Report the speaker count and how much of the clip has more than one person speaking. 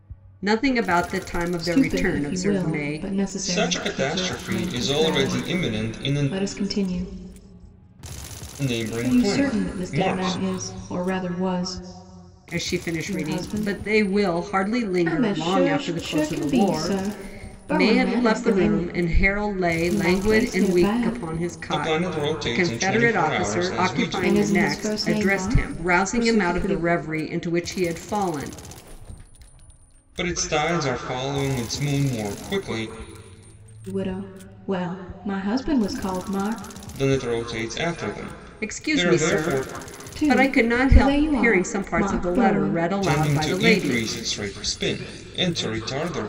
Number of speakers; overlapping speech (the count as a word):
three, about 50%